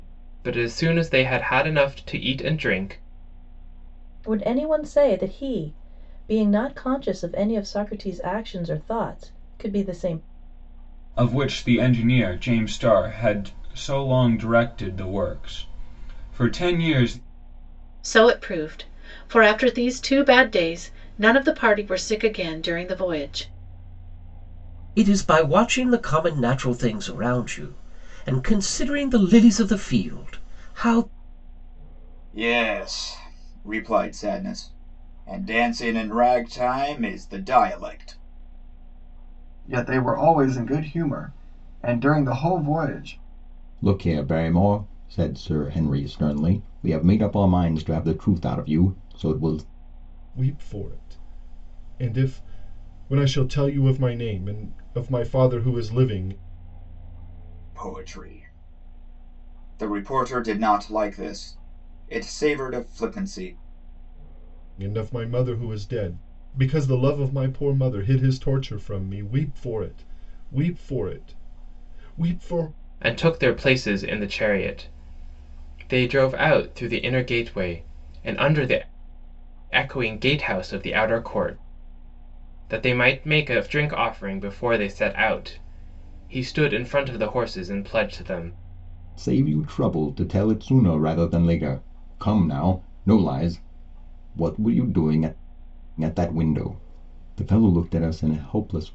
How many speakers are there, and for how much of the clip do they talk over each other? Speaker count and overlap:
9, no overlap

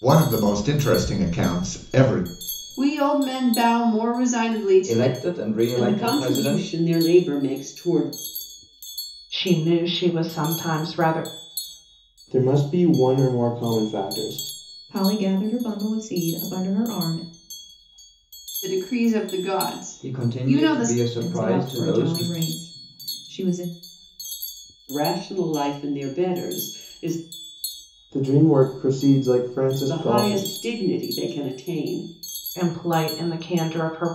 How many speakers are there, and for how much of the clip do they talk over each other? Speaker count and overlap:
7, about 12%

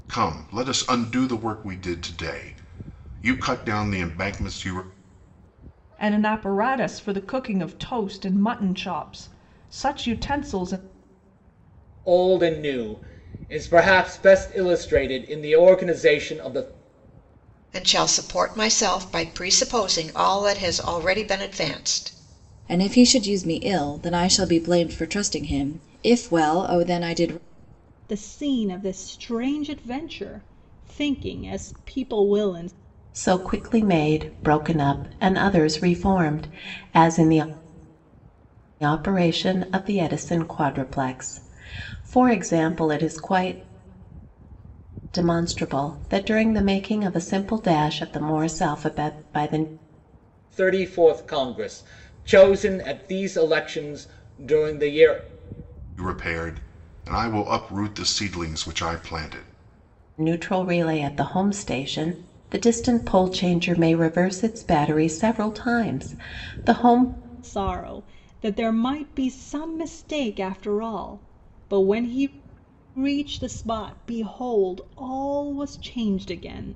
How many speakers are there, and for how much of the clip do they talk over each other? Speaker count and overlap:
7, no overlap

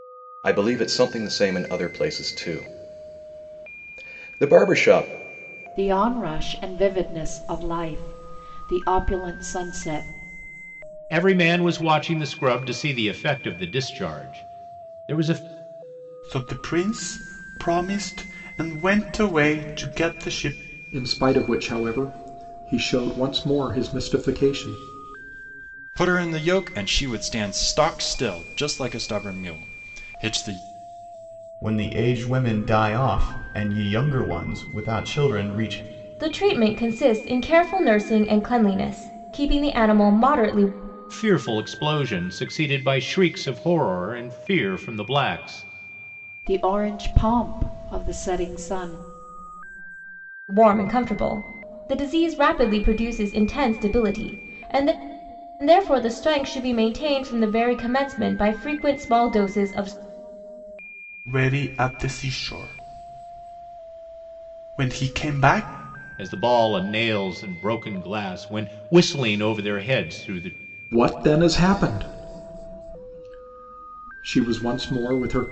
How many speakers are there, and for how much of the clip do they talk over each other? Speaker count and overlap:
8, no overlap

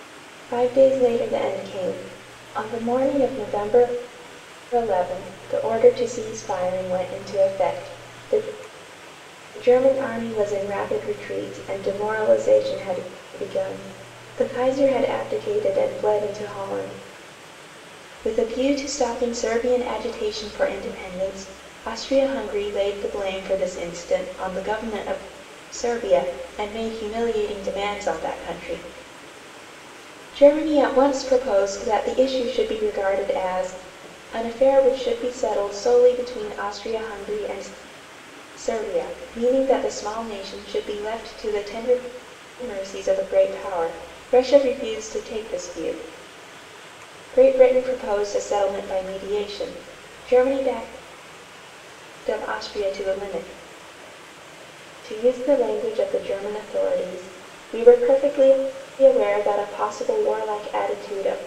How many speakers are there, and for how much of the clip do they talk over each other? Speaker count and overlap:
1, no overlap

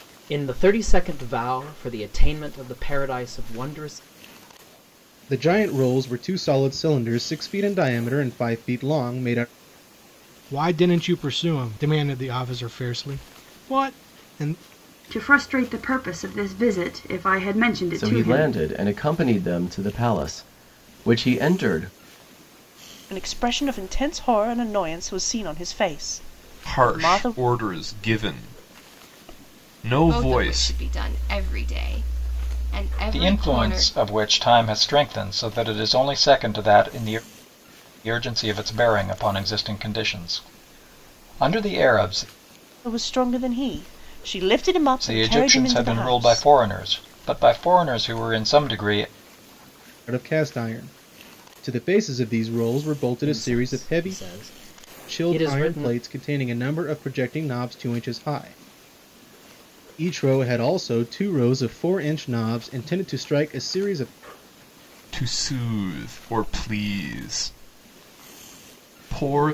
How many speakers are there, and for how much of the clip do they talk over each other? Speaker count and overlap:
9, about 9%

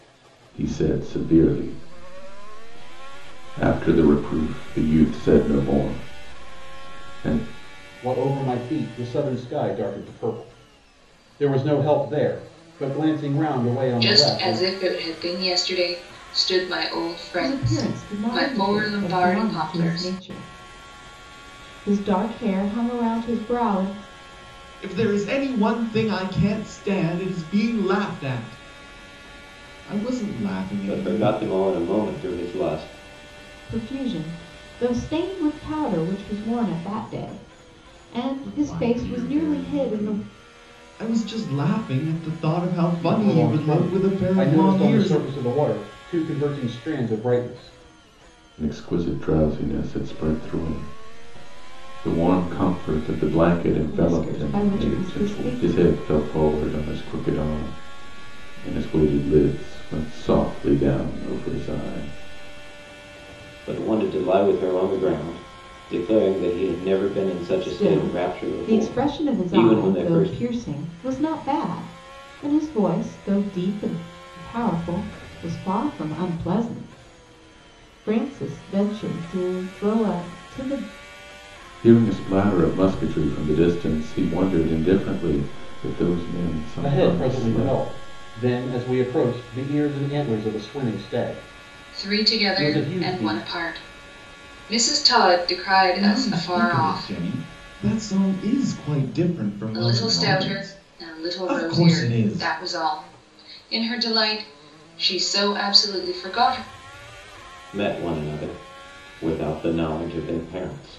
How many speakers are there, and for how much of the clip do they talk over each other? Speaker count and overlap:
6, about 18%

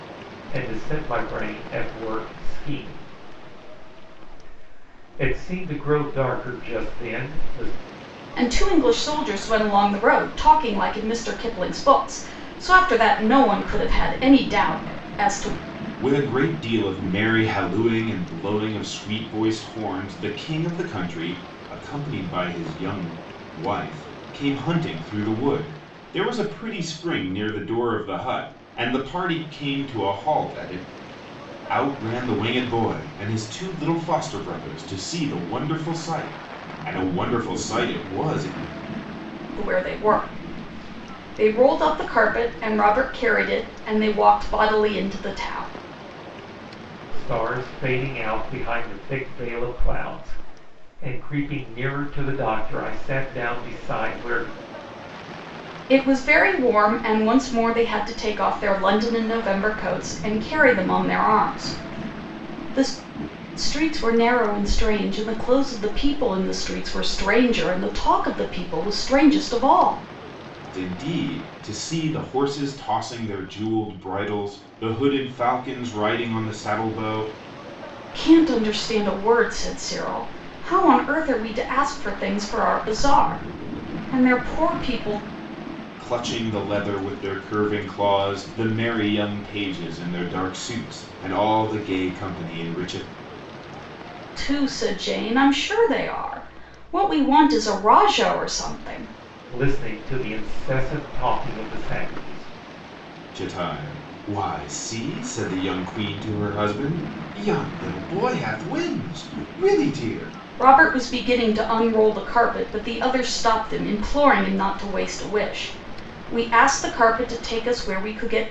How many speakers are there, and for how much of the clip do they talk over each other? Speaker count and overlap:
3, no overlap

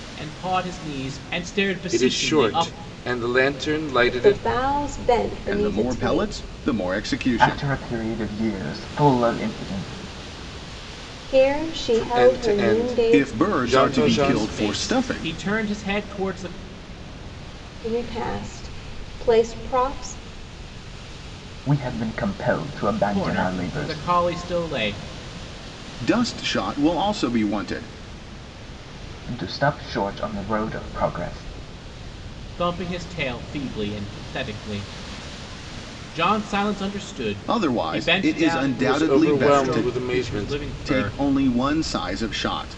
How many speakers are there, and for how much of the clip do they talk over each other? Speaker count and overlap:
5, about 25%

